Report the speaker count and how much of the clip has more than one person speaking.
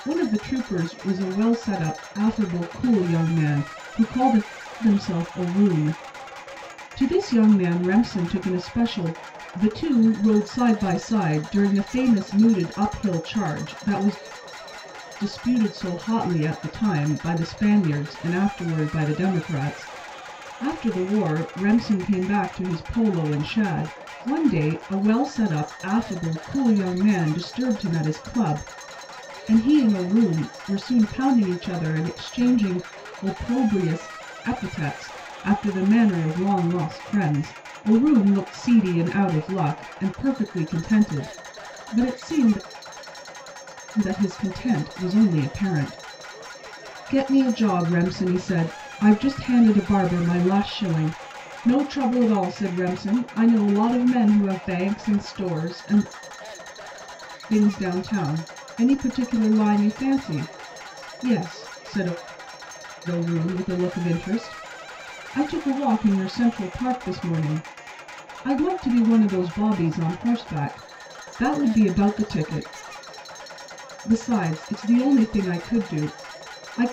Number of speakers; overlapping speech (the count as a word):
one, no overlap